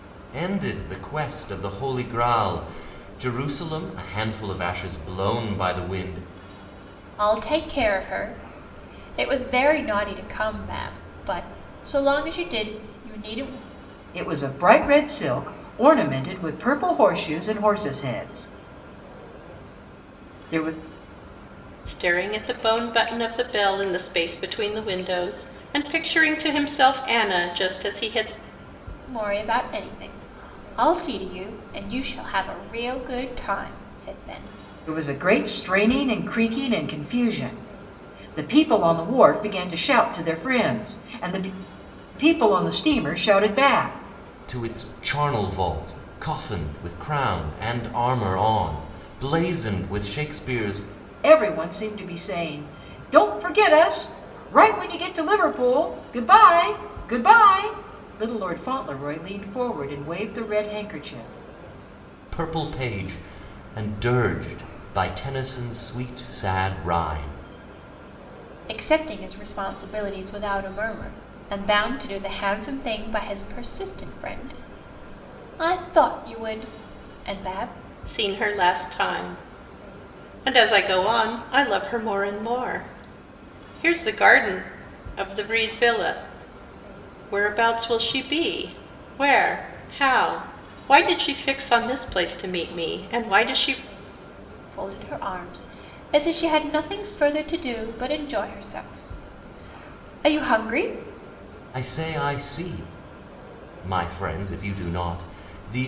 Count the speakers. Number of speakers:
4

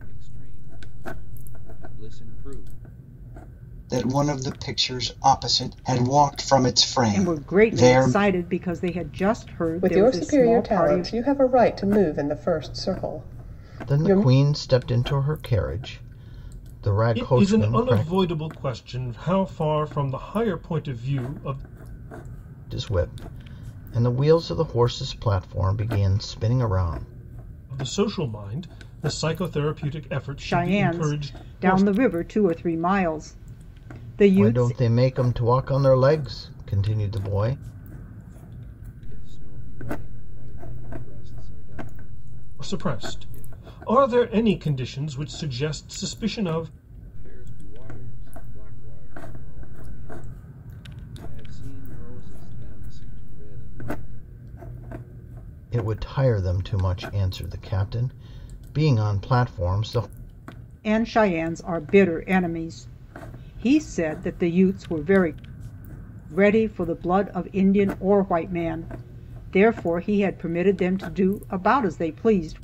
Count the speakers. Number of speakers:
6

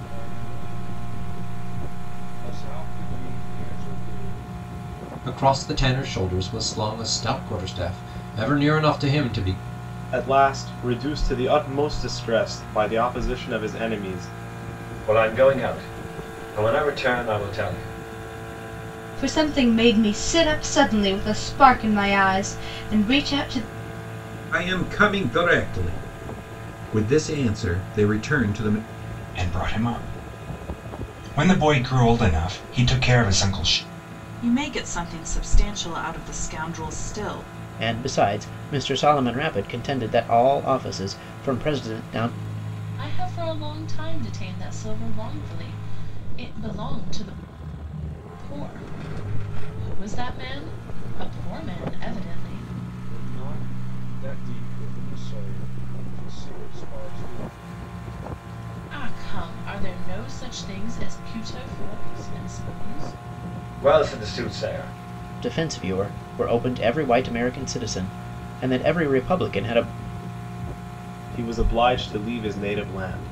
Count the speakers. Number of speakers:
10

